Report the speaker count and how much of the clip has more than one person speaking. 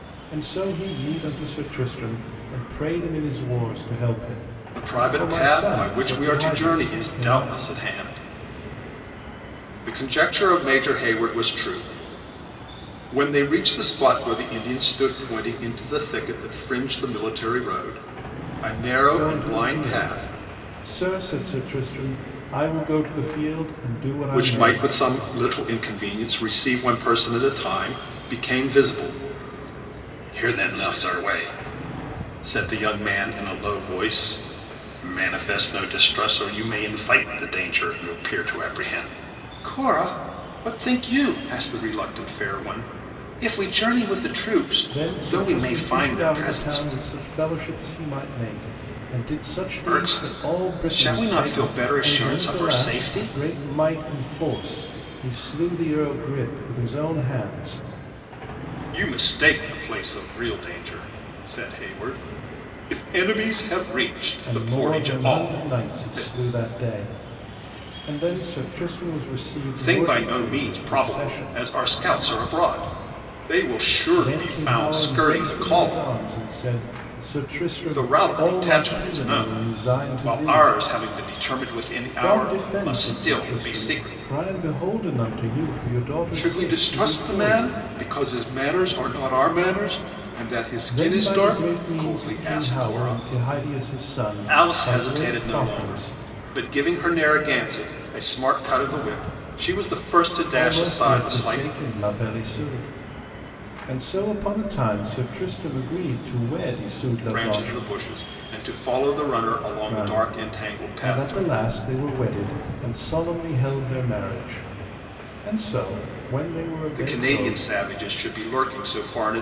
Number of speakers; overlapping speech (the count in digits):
2, about 26%